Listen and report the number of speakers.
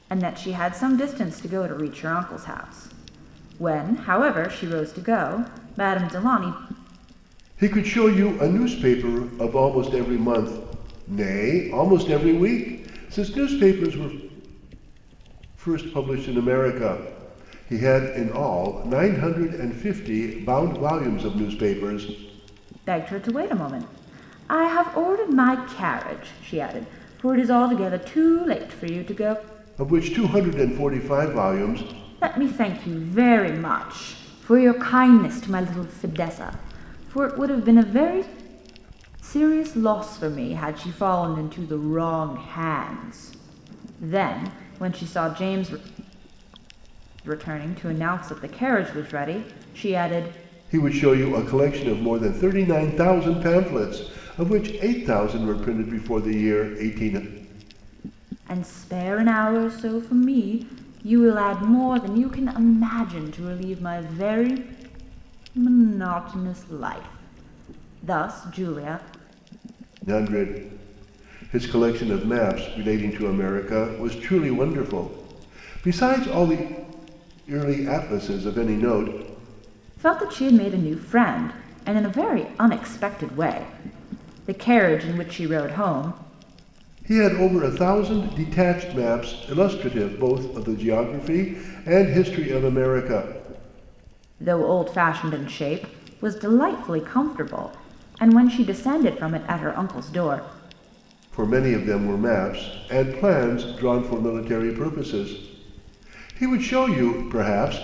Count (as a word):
two